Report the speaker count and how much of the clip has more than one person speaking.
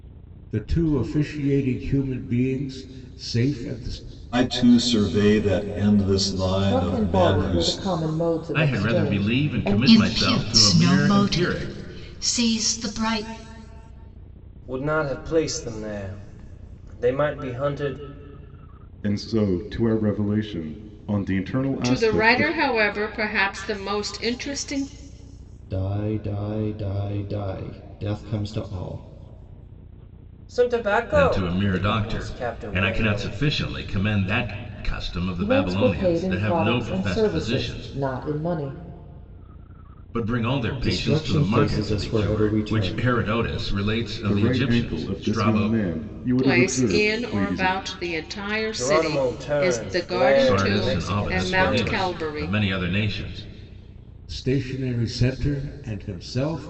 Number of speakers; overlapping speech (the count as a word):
nine, about 34%